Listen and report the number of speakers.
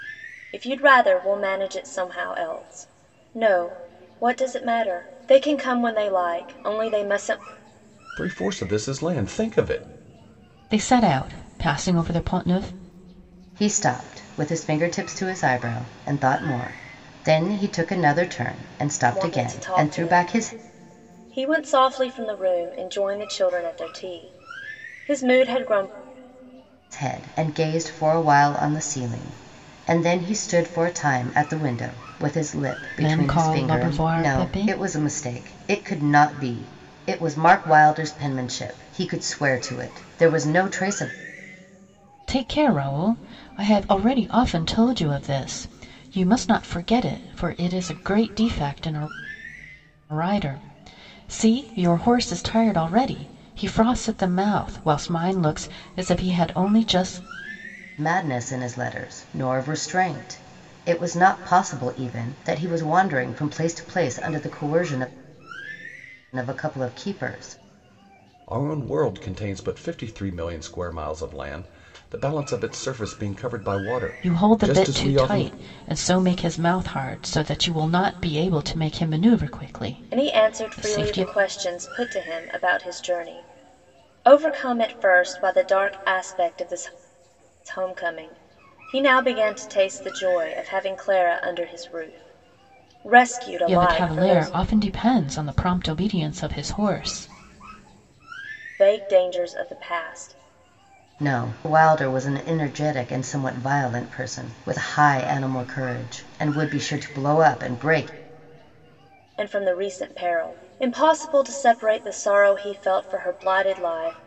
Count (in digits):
4